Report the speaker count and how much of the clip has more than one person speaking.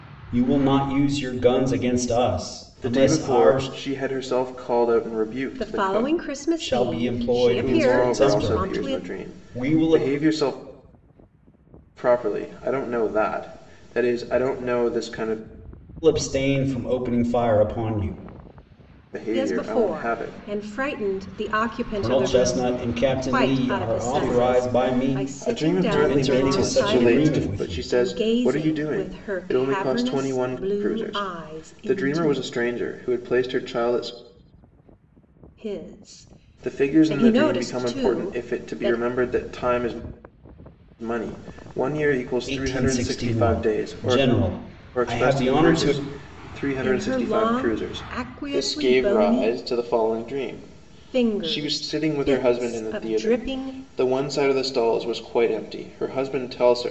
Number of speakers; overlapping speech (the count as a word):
three, about 46%